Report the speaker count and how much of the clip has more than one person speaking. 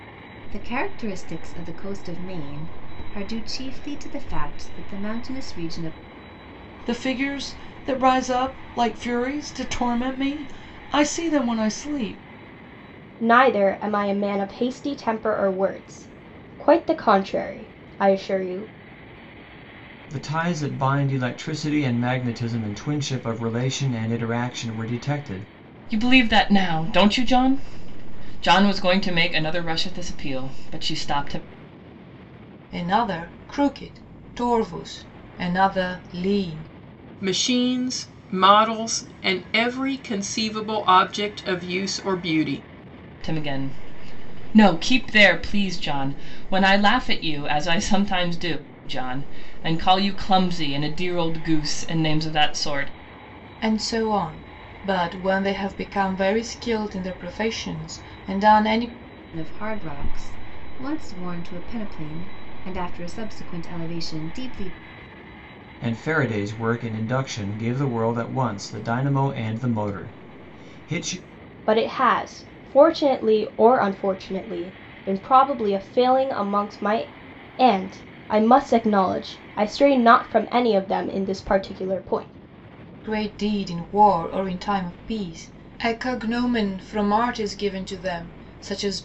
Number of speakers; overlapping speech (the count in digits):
7, no overlap